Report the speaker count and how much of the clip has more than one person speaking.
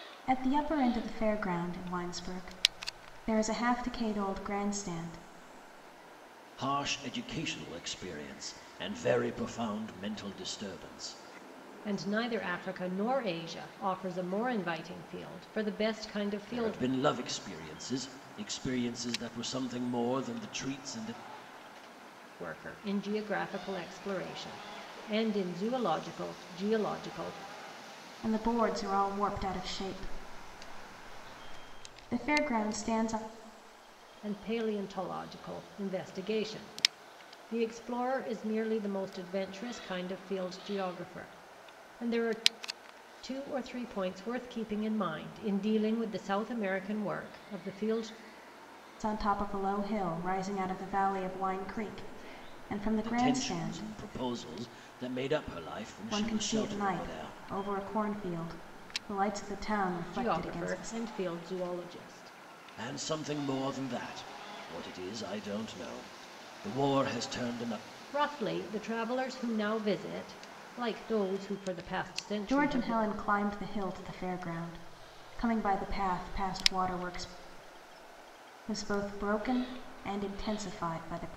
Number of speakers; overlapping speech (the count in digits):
3, about 5%